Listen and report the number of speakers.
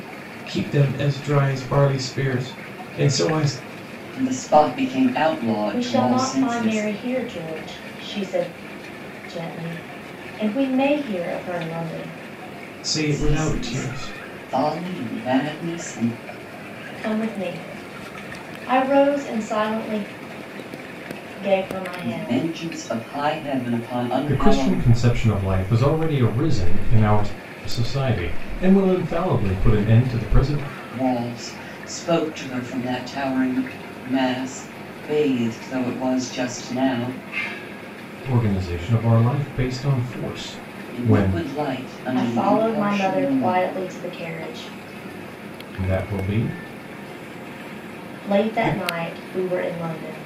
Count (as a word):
three